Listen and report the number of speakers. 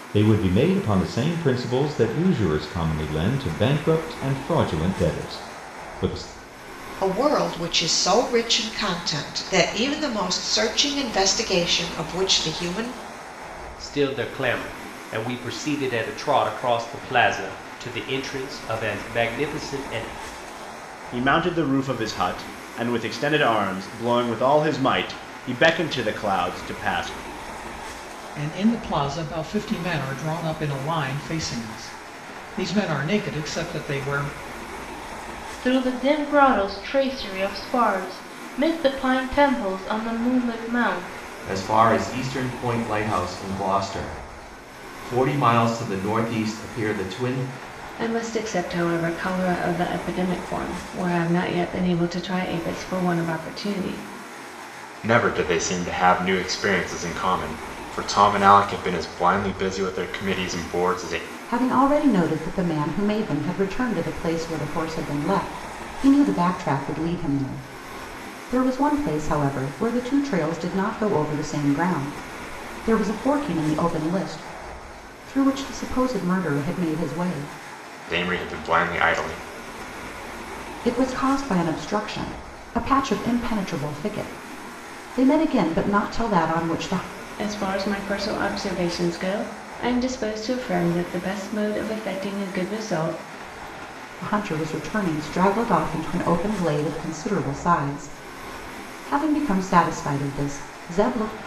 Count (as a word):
ten